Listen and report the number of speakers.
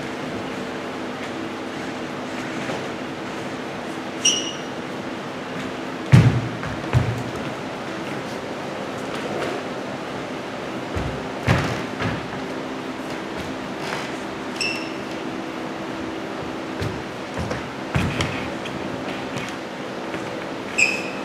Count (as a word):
zero